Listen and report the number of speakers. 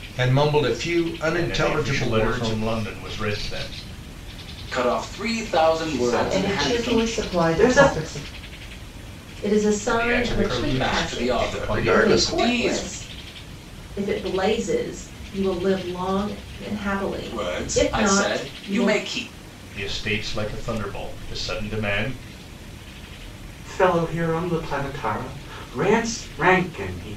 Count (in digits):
6